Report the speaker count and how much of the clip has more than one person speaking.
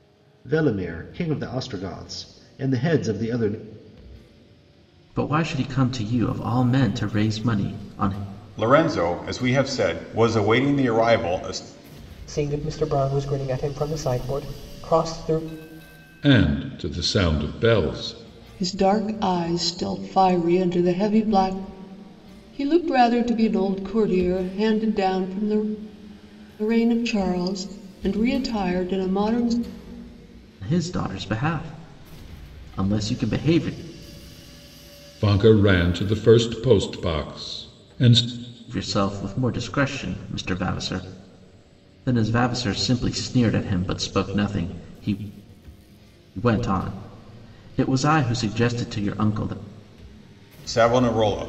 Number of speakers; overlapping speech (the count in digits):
6, no overlap